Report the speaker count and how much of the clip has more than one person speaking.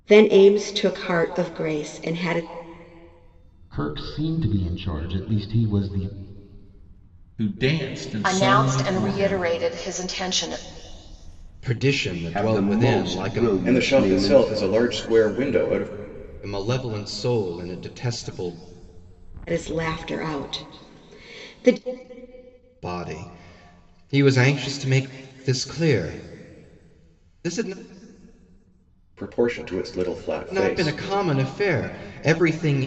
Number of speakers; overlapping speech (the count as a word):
seven, about 12%